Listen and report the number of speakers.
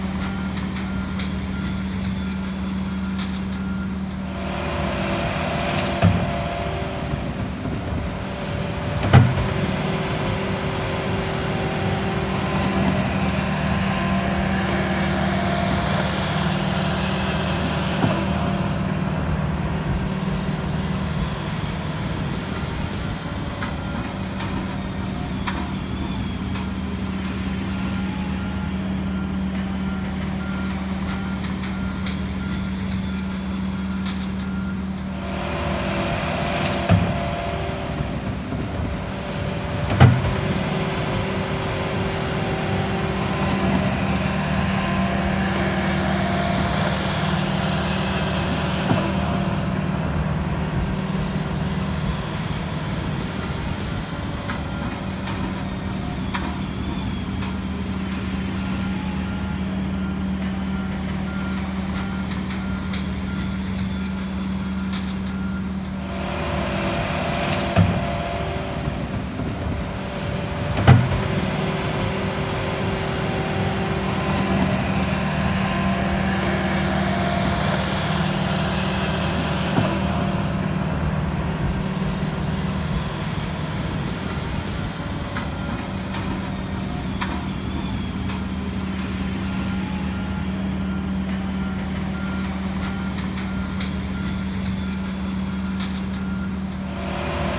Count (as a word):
zero